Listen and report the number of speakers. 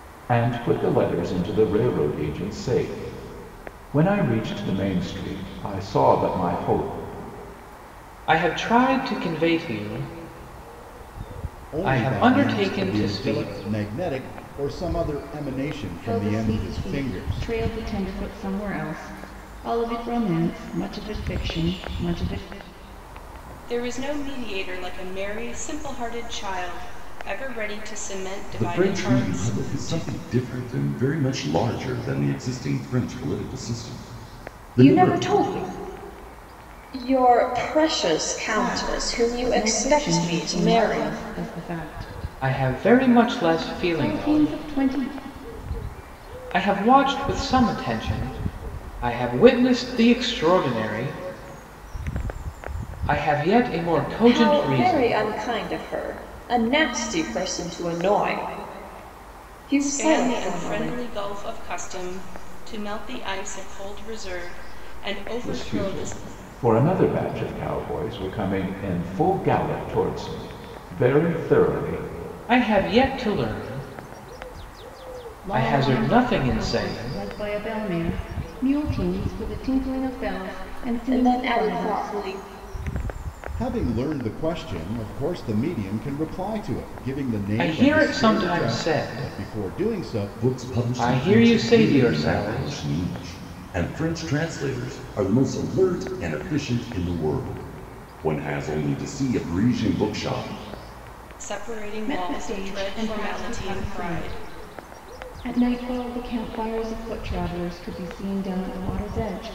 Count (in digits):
7